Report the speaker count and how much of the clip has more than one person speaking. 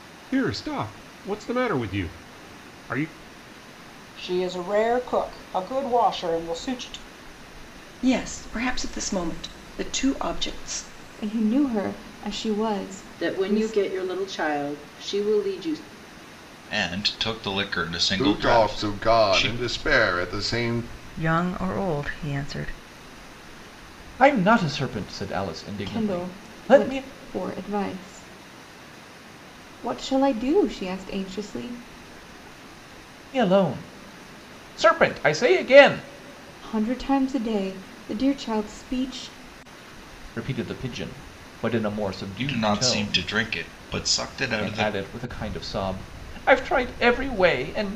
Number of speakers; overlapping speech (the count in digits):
9, about 10%